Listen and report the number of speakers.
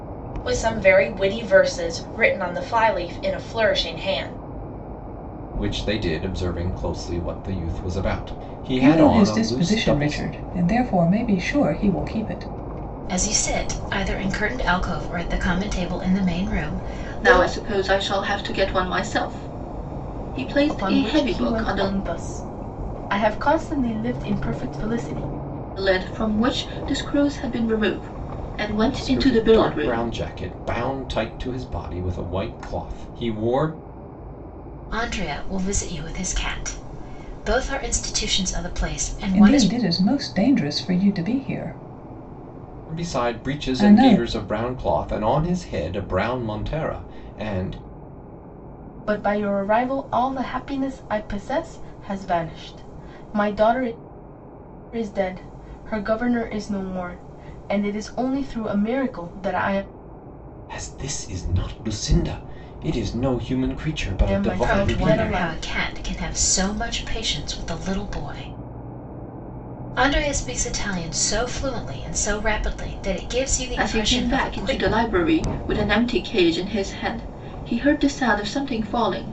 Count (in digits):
6